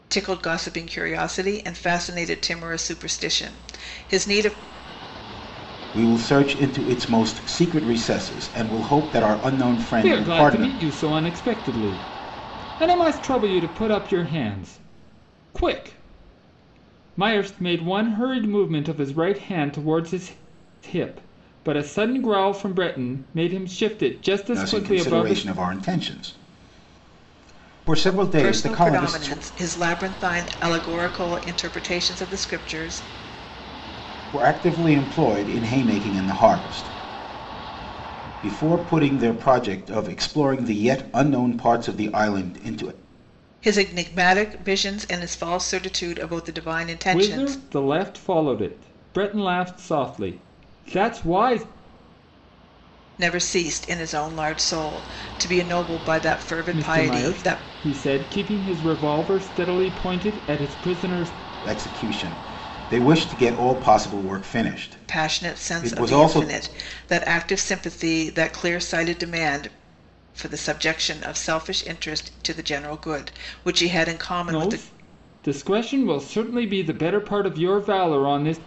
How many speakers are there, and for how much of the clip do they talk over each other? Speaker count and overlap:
3, about 8%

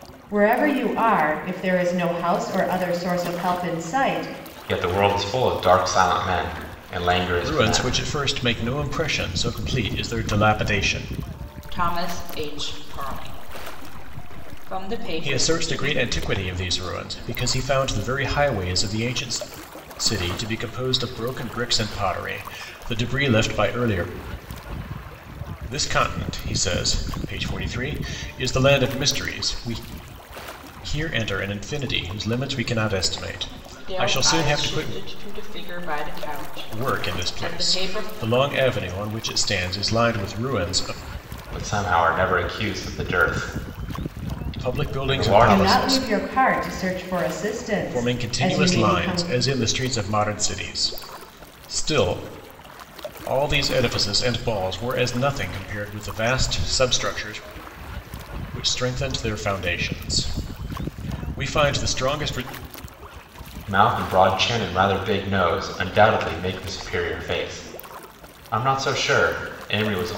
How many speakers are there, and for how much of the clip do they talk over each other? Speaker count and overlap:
4, about 10%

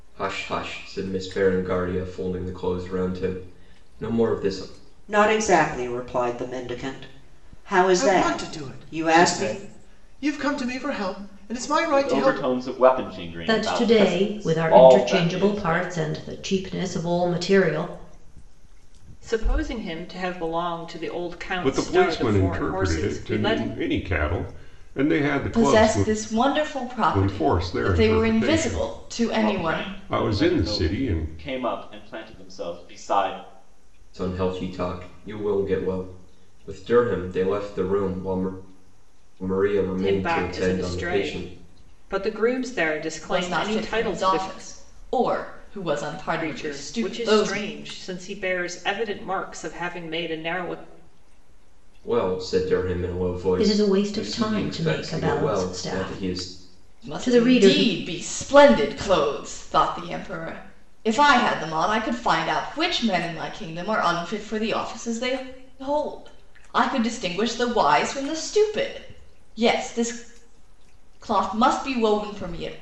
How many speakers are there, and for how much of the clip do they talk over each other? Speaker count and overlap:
8, about 27%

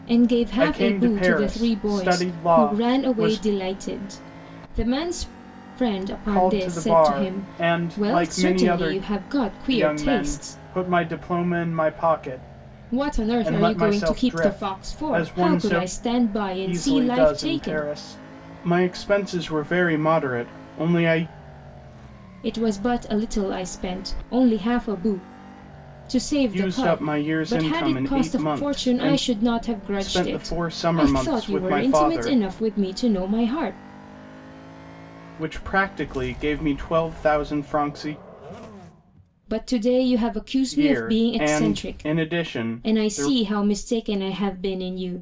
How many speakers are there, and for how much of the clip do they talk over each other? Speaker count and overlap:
2, about 38%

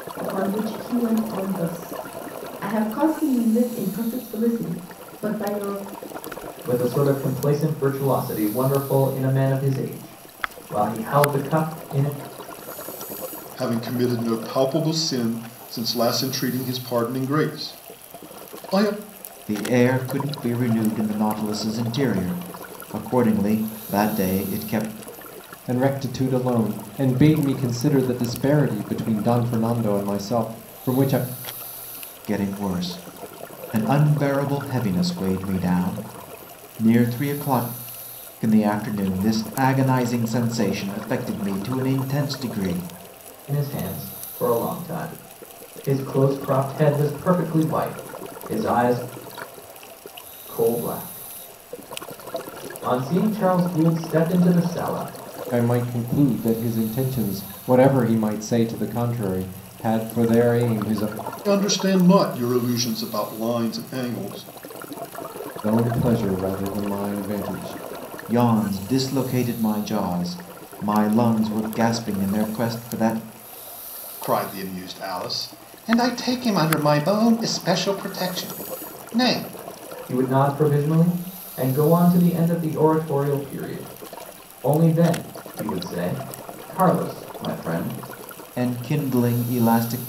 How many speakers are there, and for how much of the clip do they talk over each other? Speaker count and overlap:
5, no overlap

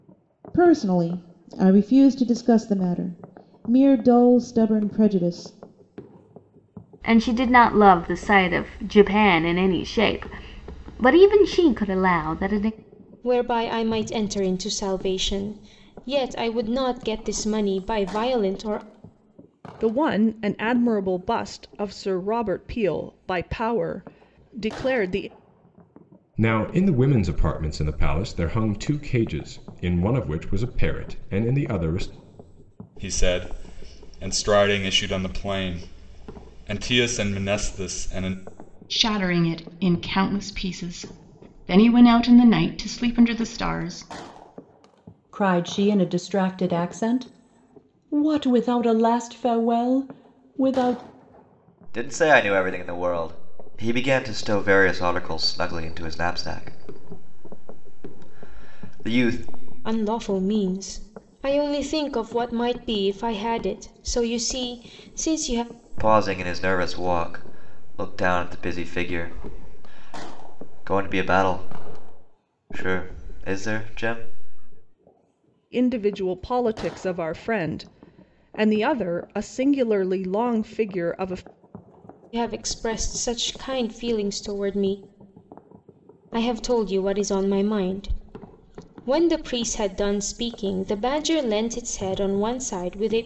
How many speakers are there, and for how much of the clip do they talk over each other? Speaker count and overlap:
9, no overlap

